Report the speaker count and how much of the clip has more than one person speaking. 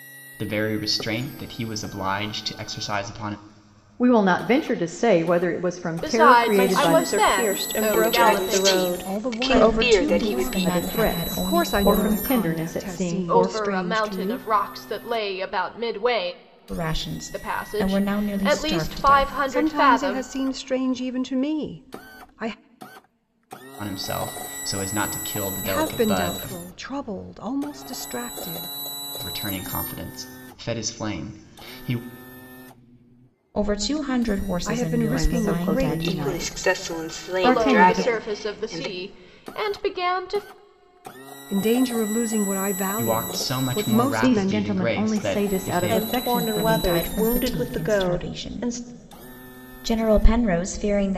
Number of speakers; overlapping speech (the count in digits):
7, about 44%